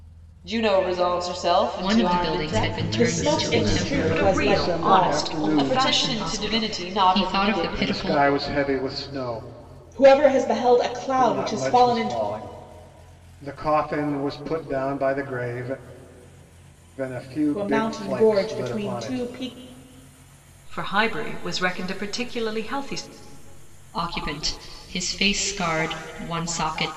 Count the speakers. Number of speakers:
6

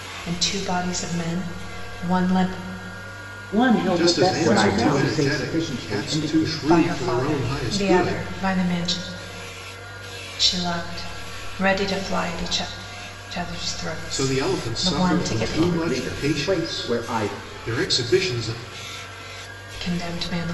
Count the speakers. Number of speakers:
4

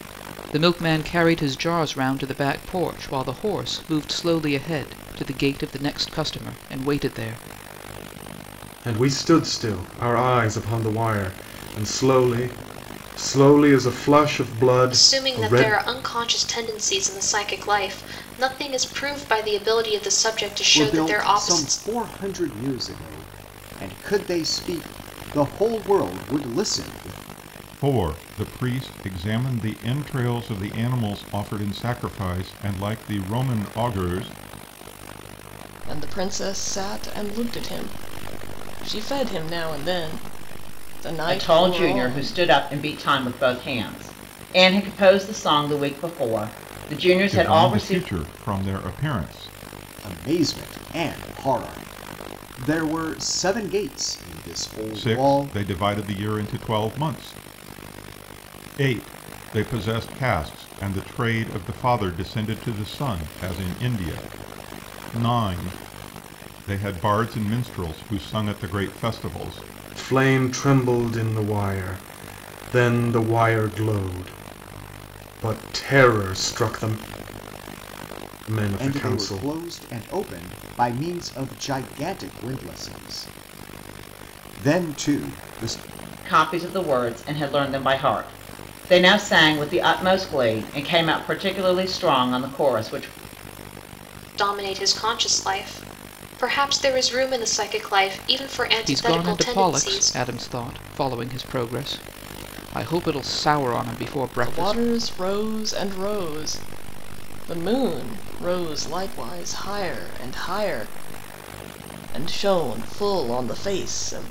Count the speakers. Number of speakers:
7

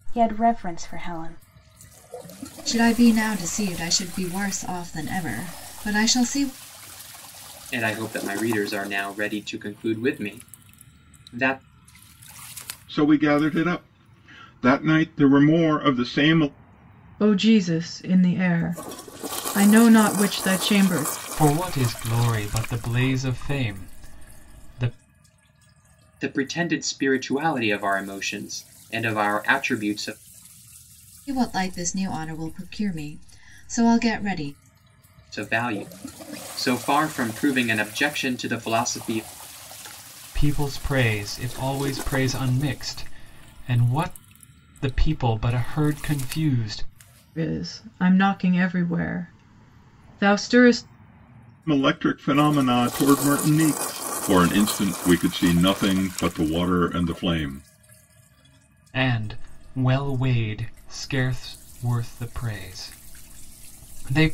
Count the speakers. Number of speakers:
6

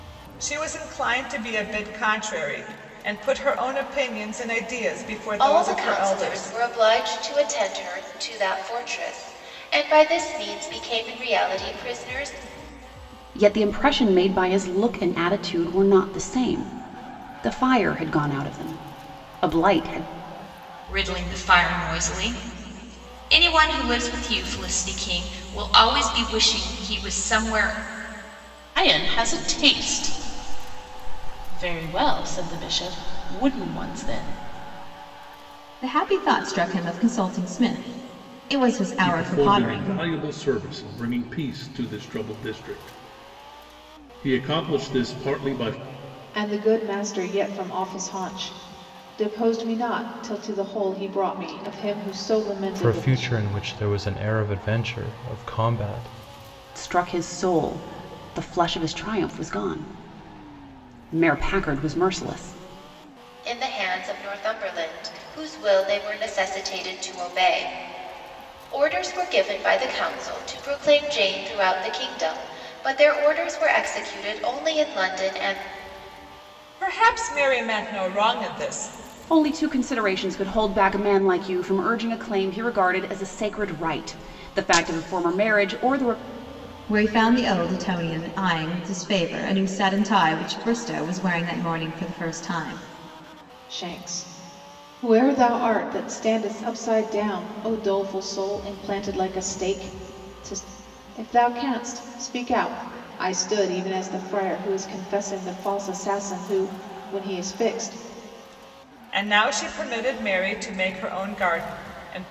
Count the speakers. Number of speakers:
9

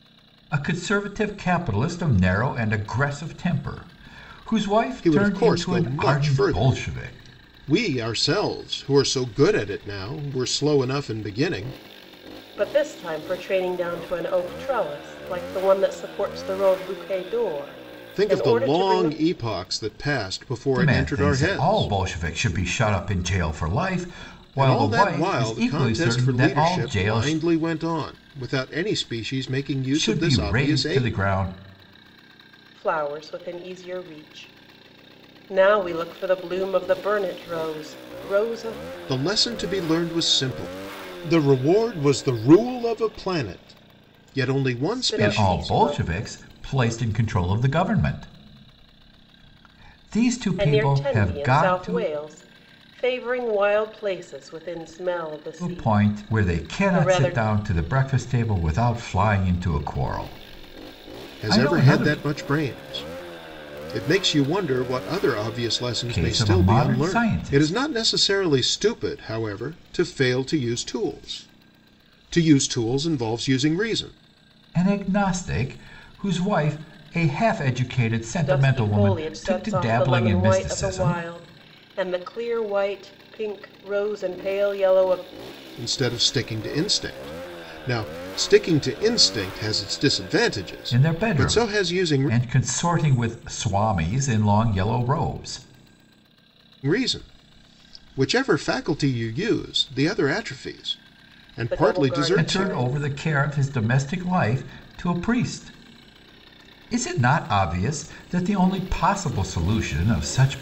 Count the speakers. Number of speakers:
3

